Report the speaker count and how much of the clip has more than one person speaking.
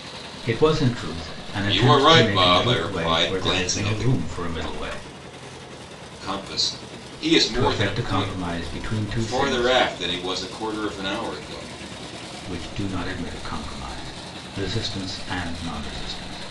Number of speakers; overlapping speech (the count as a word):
two, about 24%